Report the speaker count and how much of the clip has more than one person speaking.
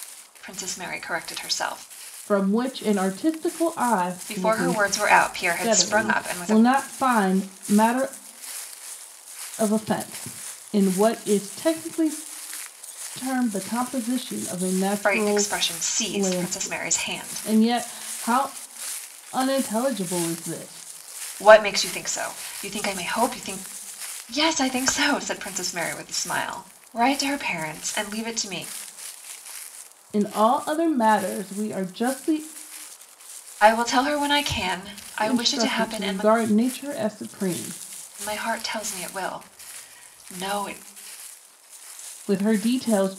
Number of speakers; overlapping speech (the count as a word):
two, about 11%